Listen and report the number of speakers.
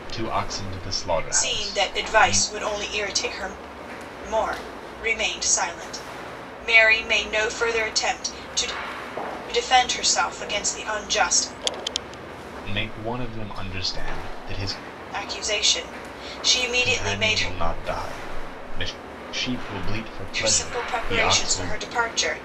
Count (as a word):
two